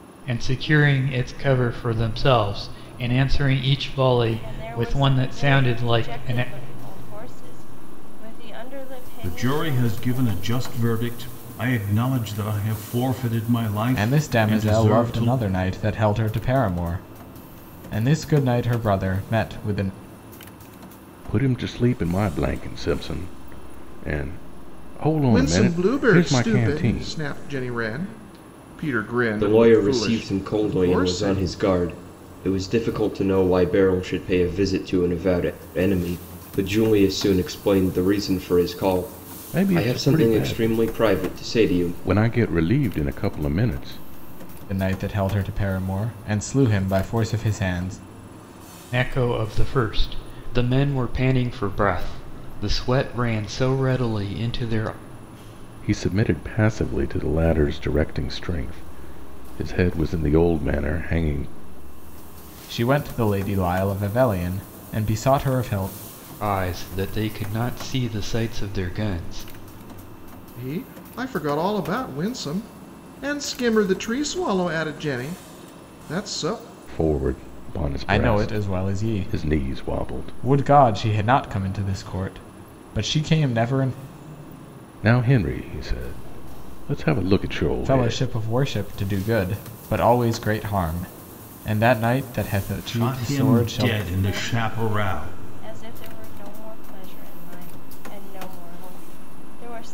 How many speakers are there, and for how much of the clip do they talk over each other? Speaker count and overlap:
7, about 17%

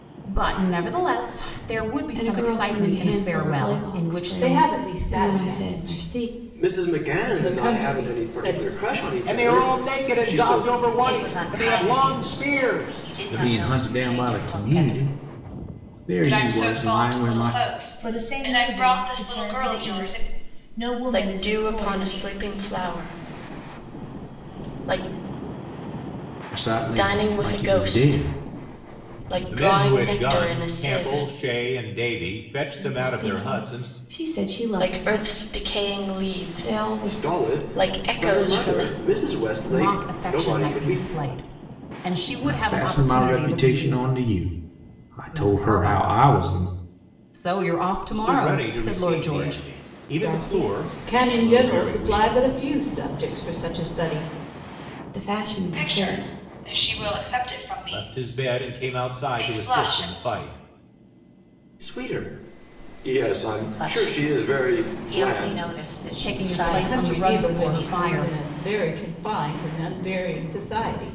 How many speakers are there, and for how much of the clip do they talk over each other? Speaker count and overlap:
10, about 57%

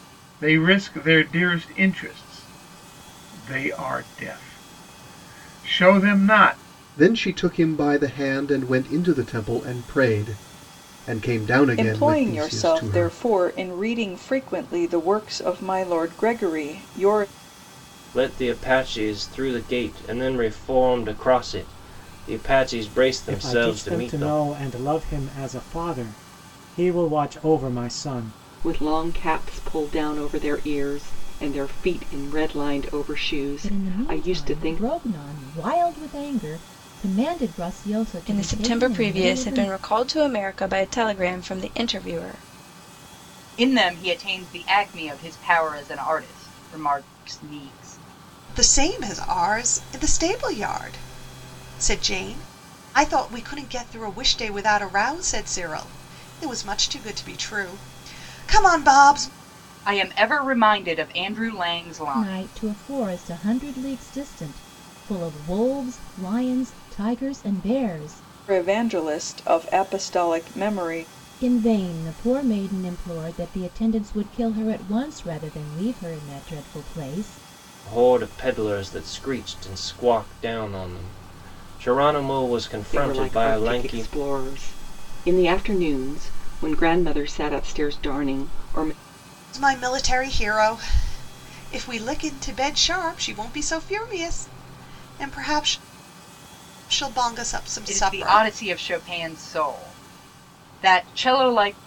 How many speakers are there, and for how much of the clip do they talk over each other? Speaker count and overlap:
10, about 8%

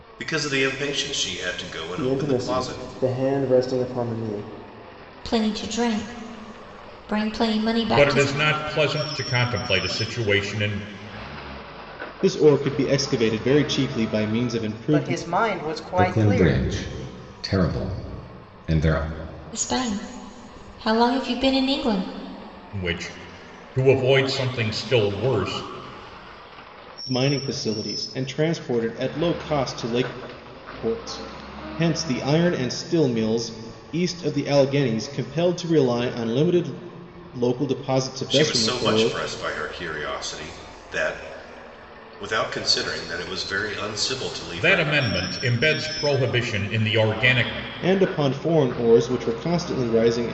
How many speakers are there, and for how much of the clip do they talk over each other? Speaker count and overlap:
7, about 7%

